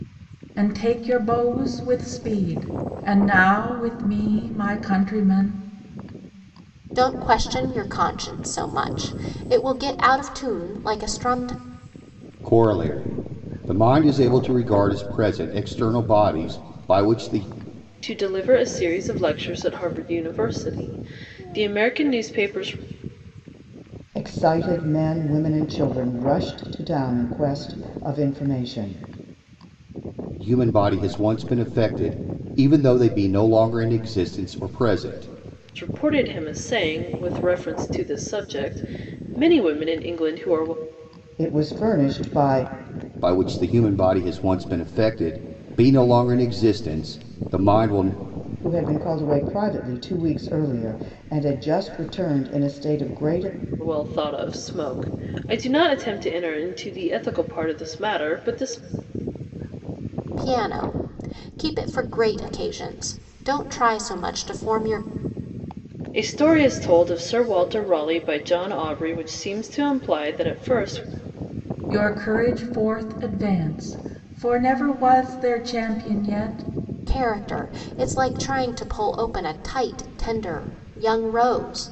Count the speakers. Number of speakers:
5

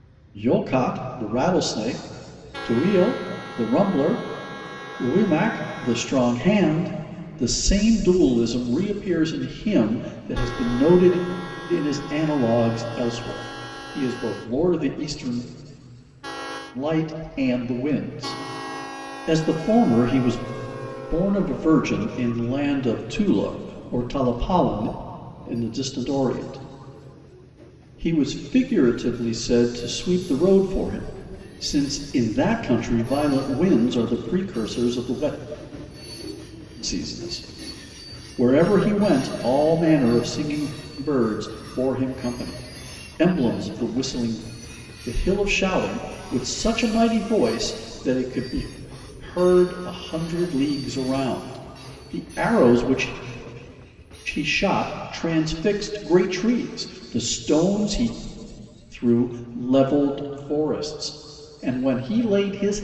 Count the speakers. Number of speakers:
1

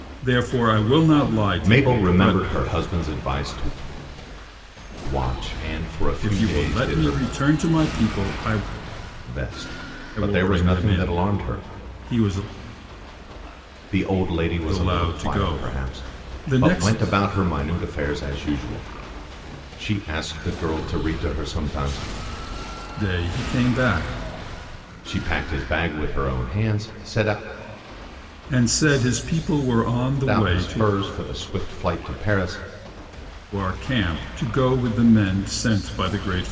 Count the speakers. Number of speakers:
2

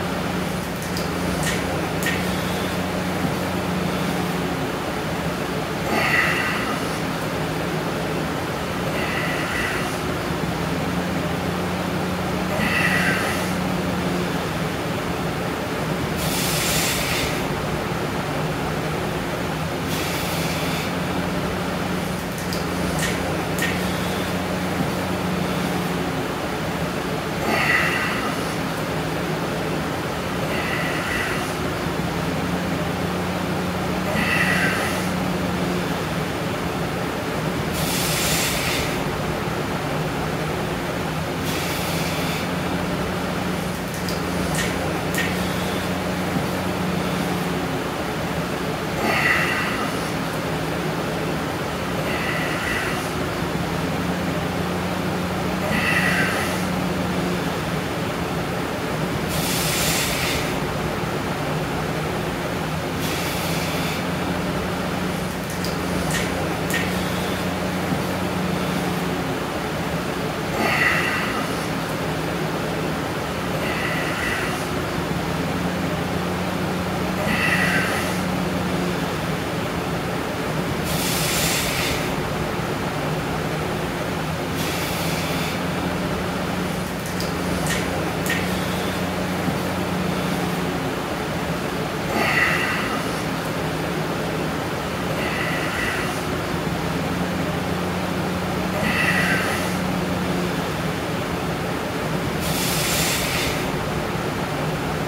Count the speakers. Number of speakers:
0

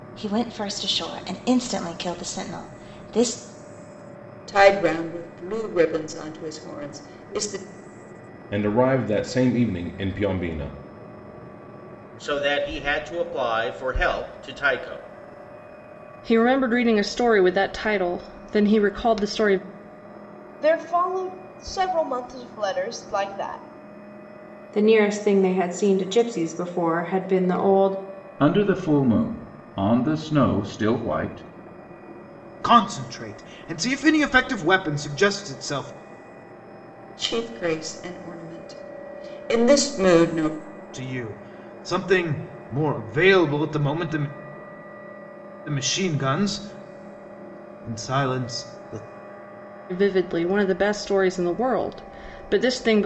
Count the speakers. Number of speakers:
9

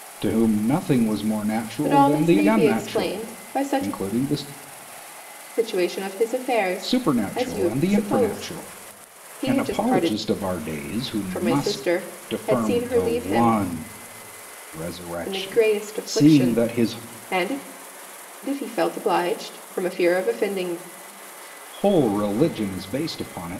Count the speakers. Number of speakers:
2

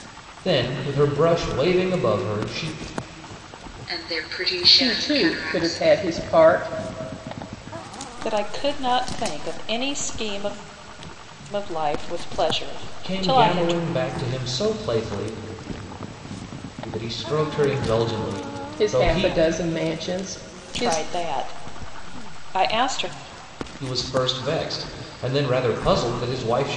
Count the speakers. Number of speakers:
4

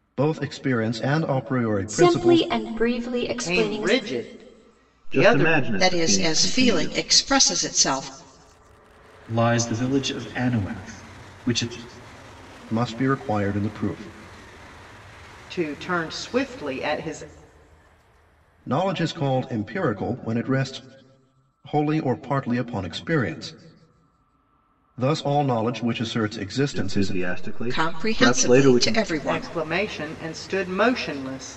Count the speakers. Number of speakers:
6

